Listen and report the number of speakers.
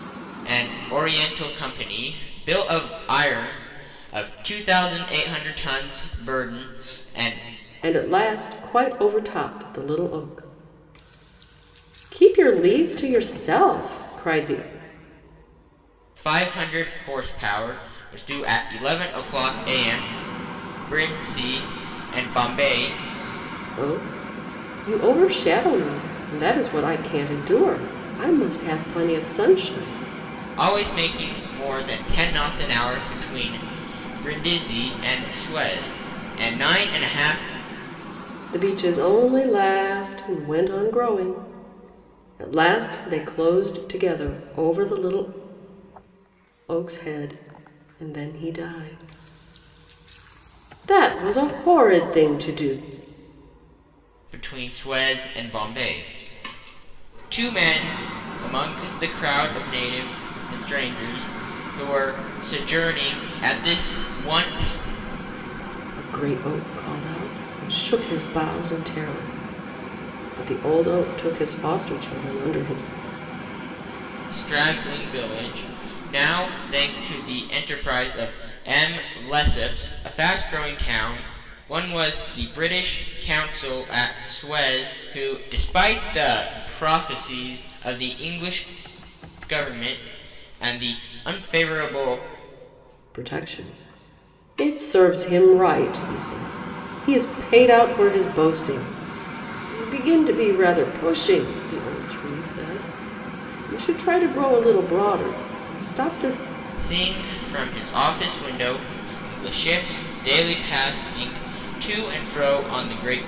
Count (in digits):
2